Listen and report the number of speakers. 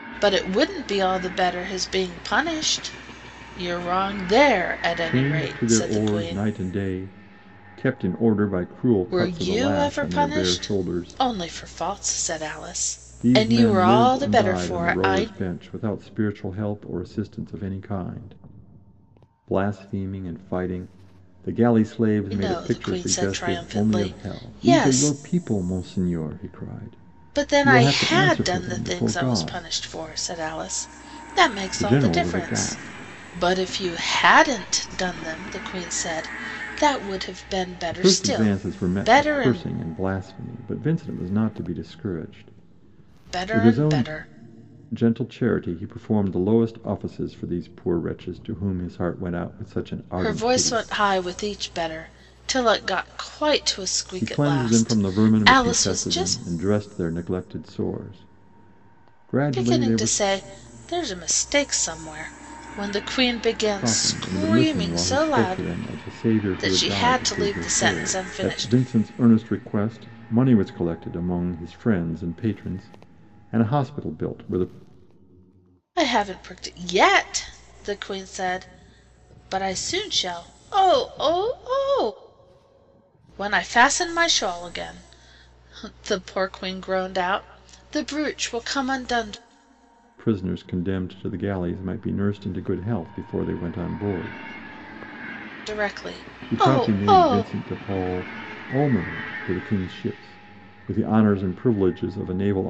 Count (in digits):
2